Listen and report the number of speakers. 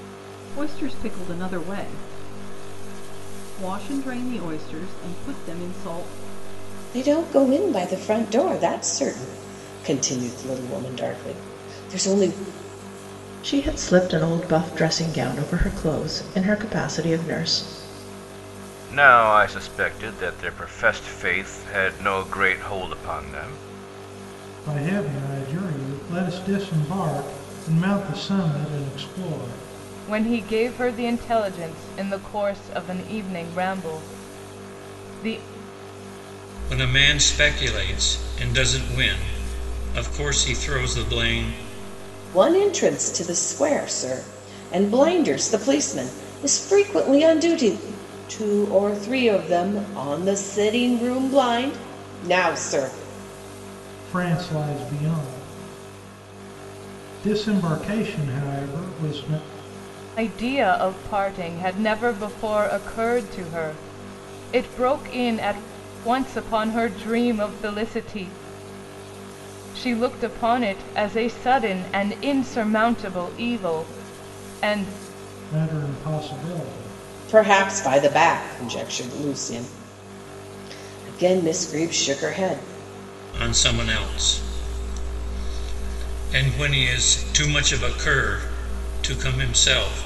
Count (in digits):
7